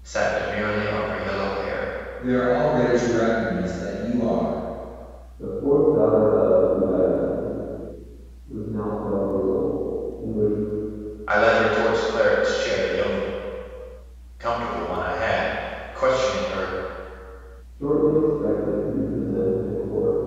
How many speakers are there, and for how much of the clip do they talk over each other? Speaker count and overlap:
three, no overlap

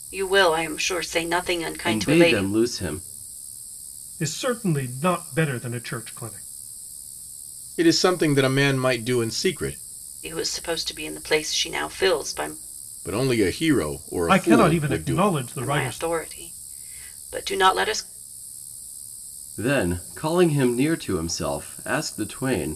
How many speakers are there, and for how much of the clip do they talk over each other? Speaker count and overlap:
four, about 9%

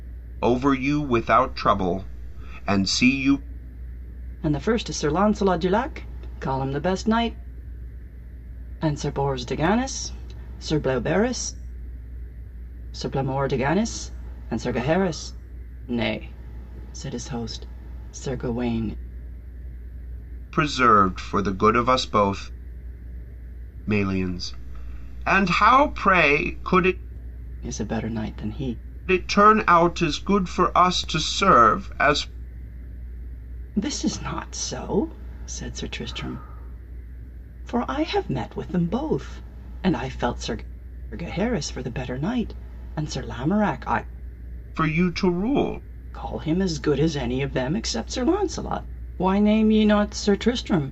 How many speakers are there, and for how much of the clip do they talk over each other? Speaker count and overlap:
two, no overlap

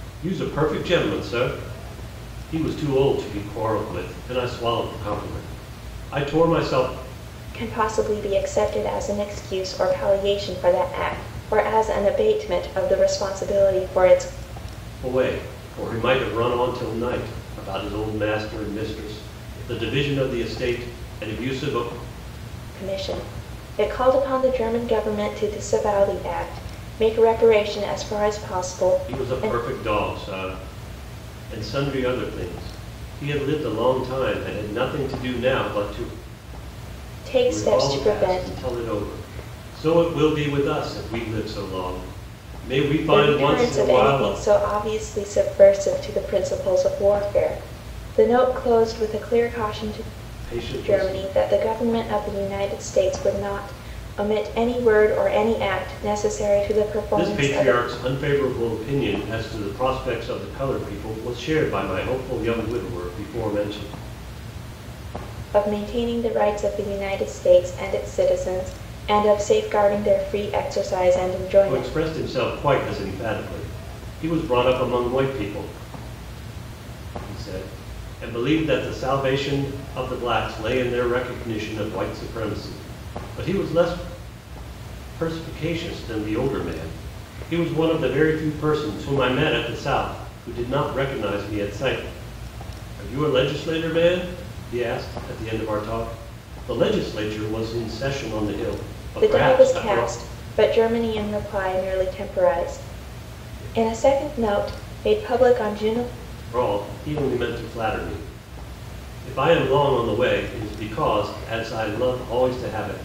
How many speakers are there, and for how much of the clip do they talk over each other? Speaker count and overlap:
two, about 5%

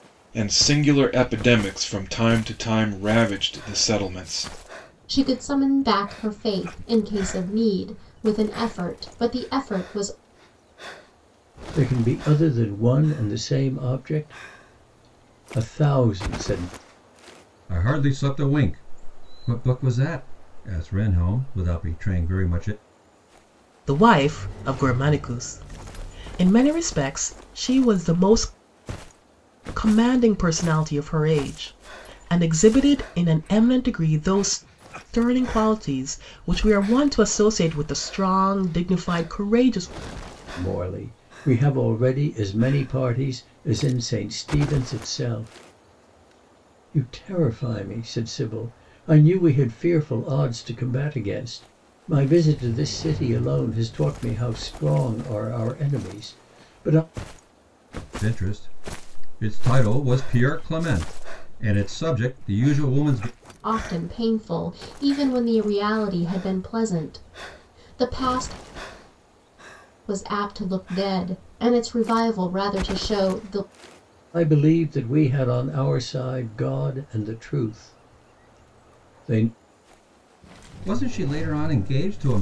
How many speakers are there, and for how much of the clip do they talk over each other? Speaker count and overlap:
five, no overlap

